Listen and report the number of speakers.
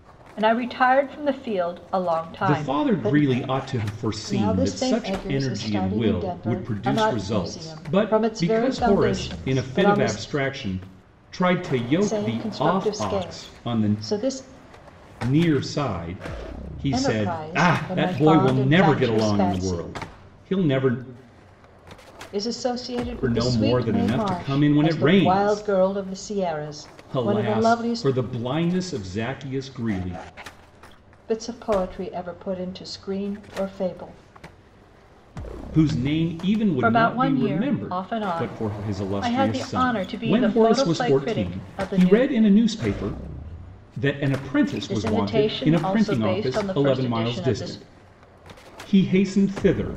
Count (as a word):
two